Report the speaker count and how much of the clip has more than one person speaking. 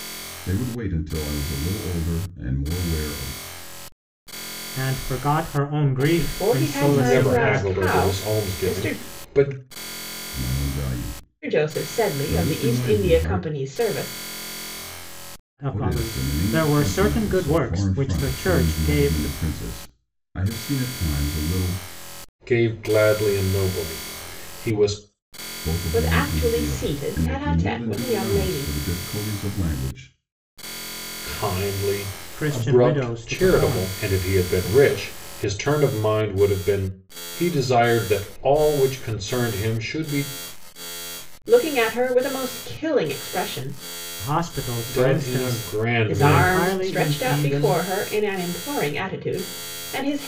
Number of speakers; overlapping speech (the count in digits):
4, about 33%